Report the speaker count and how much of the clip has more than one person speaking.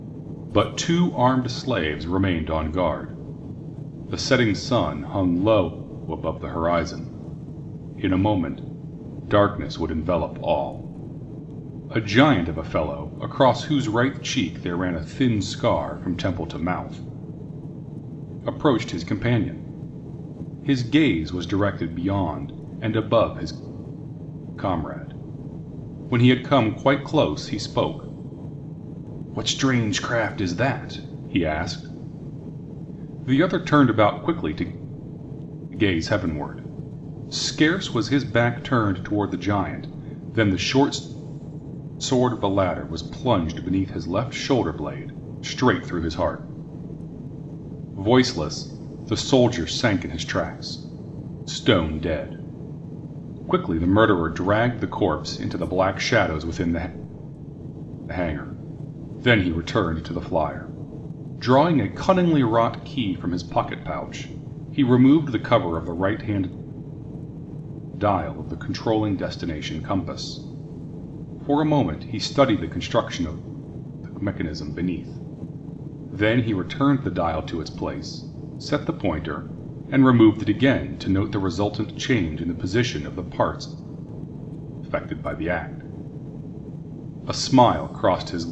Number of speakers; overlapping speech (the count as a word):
one, no overlap